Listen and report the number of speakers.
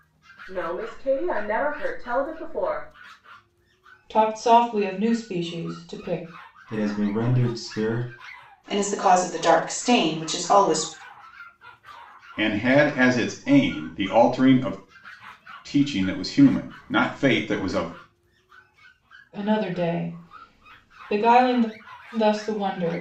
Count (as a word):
five